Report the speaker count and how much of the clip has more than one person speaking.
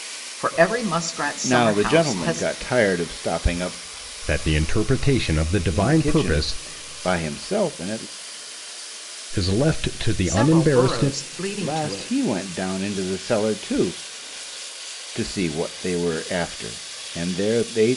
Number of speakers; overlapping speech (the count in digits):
3, about 19%